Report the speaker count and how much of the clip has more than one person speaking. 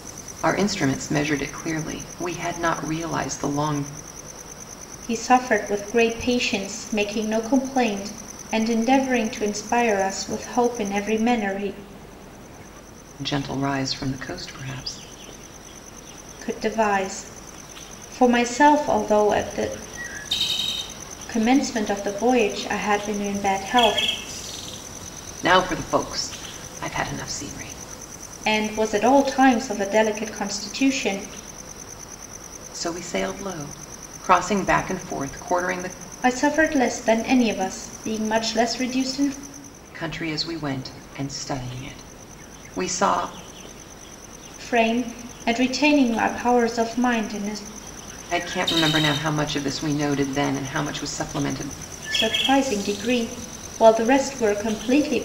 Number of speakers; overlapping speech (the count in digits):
2, no overlap